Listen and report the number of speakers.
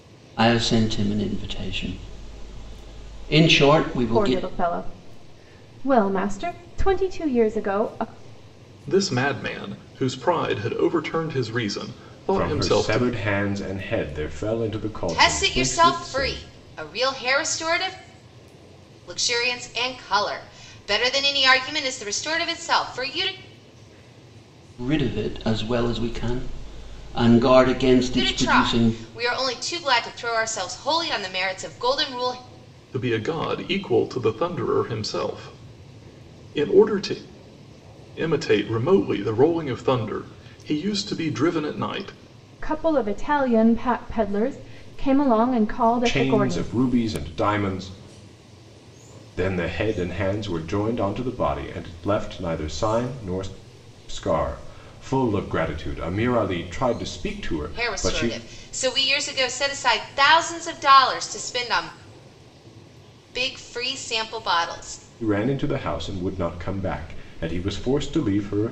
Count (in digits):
5